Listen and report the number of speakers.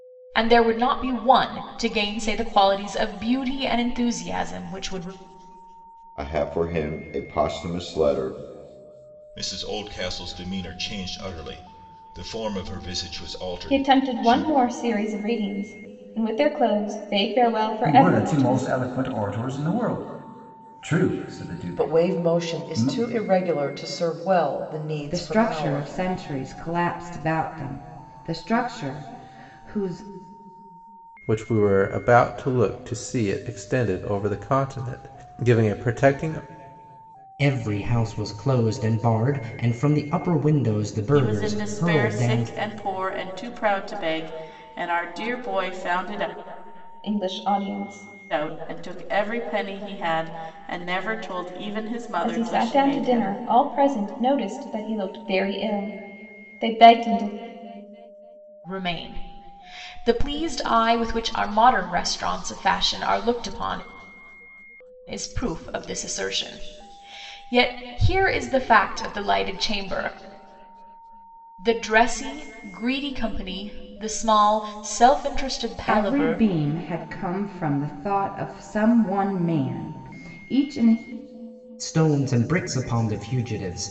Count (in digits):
10